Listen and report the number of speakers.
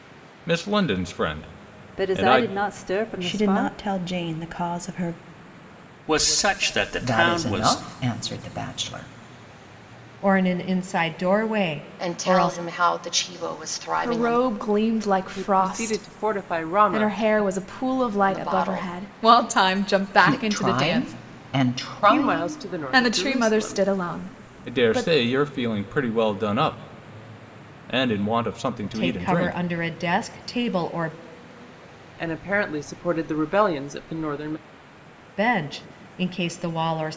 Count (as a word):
nine